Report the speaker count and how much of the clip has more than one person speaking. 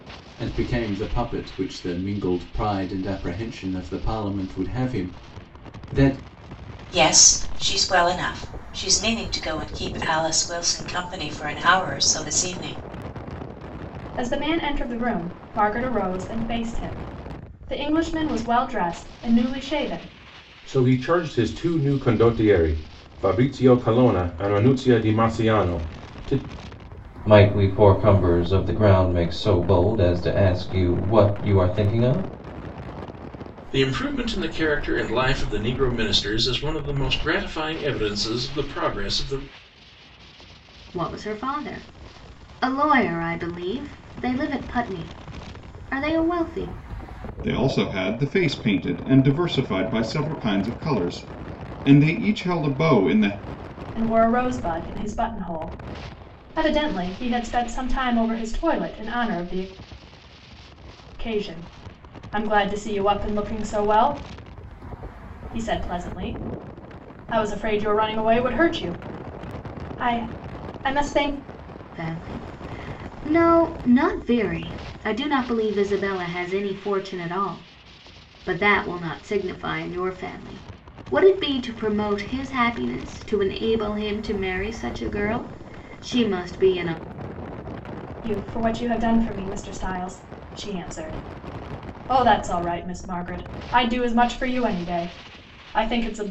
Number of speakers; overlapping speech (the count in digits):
8, no overlap